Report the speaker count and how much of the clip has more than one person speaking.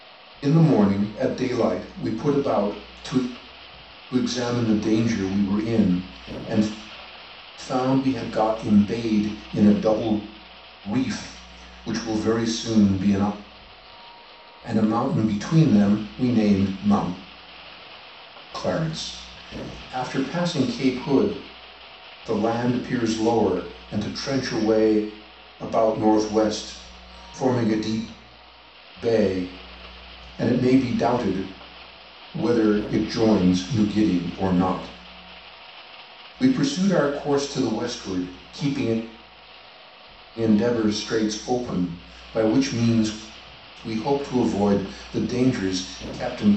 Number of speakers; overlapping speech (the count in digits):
1, no overlap